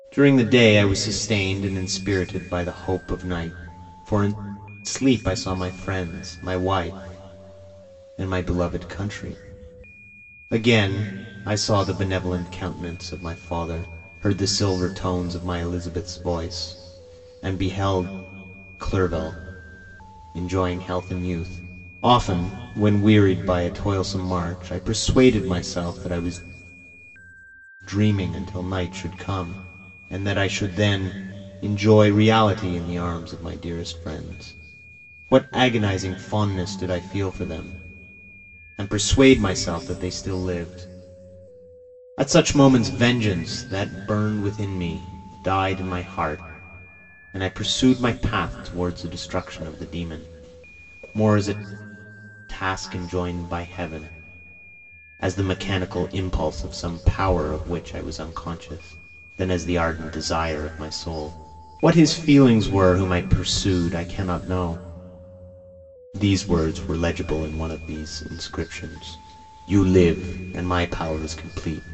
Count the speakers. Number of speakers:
1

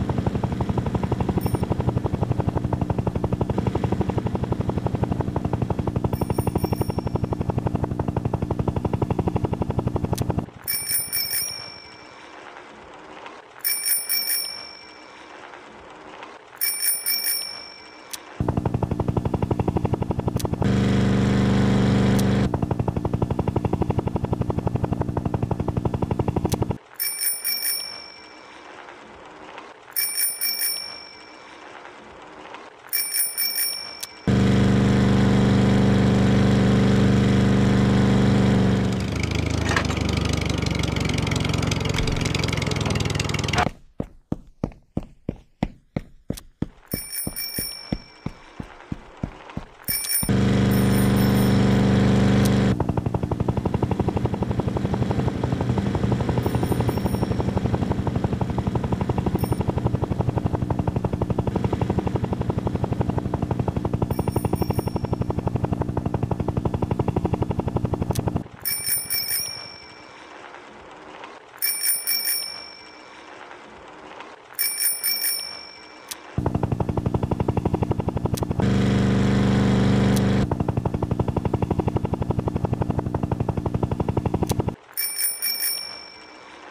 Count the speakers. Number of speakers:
0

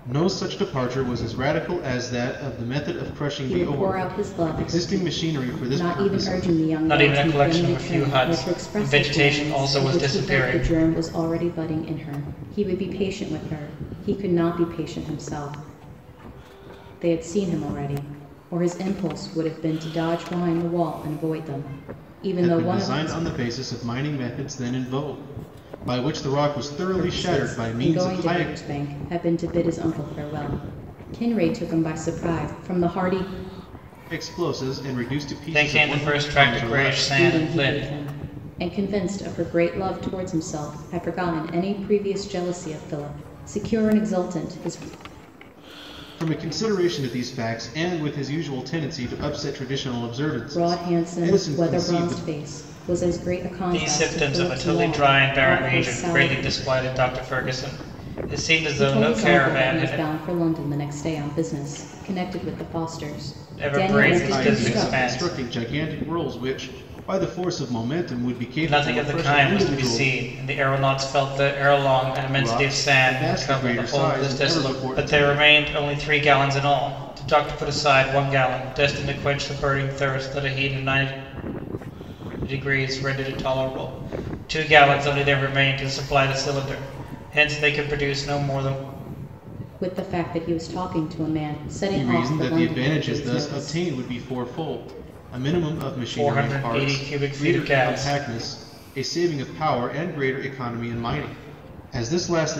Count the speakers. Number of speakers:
3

